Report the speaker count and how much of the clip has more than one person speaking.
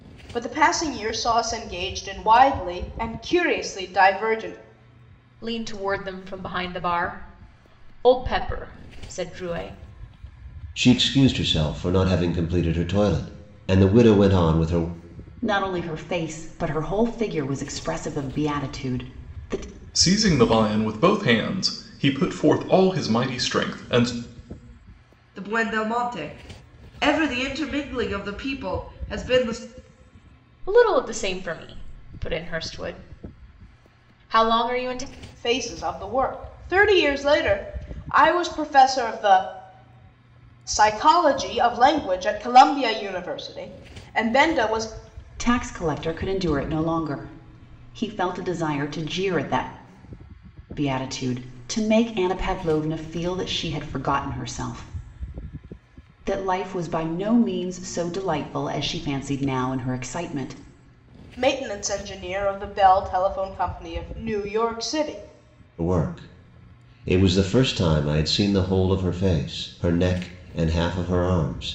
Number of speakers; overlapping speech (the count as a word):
six, no overlap